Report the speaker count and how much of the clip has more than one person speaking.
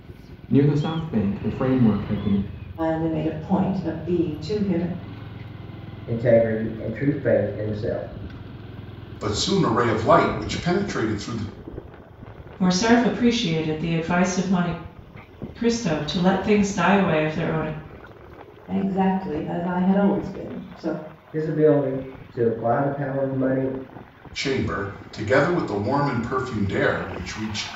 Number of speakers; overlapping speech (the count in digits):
5, no overlap